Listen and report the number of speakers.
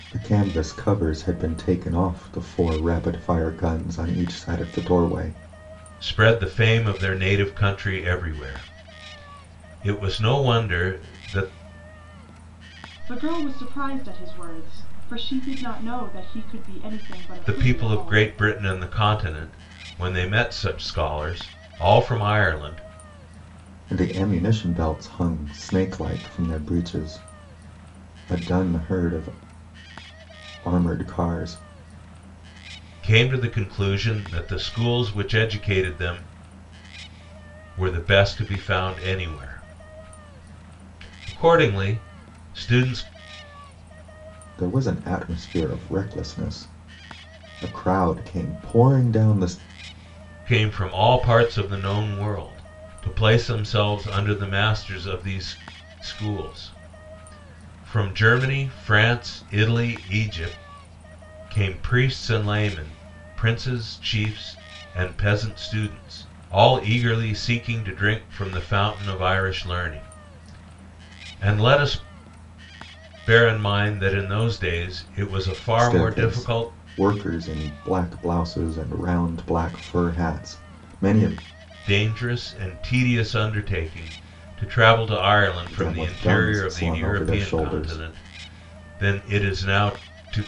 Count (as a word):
three